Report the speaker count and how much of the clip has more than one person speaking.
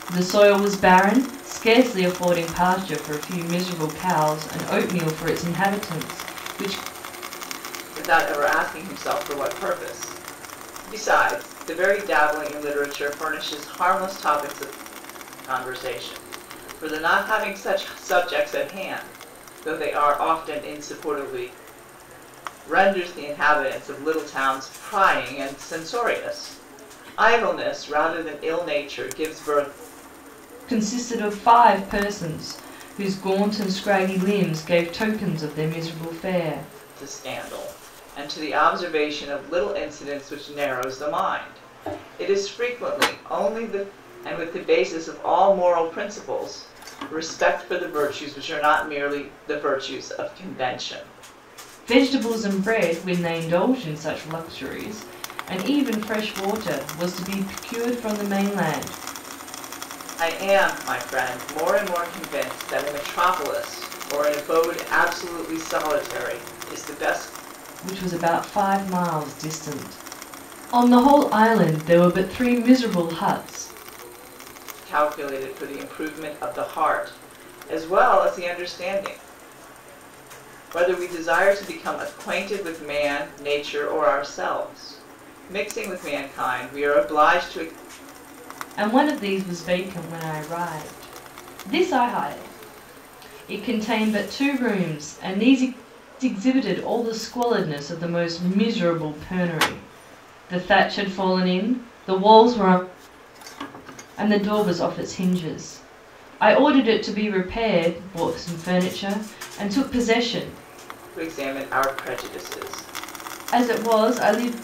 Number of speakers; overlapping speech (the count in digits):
2, no overlap